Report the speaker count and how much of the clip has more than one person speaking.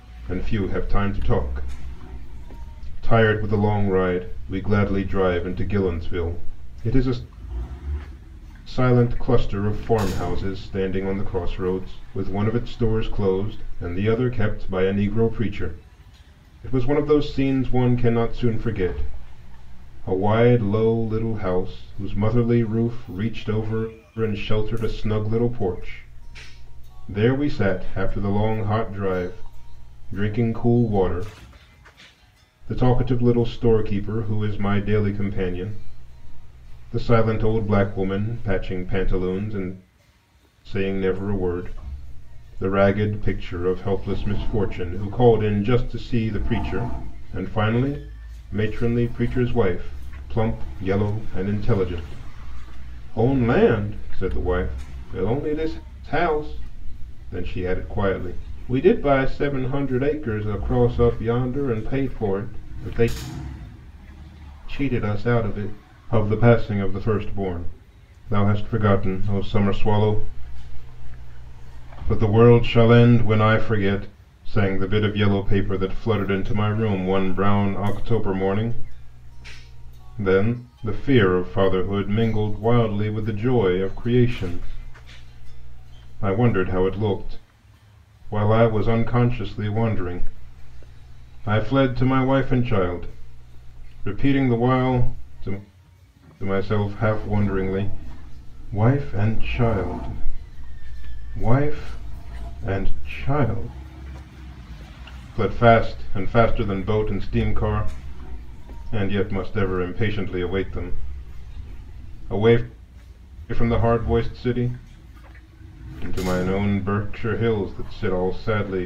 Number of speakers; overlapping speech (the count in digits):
1, no overlap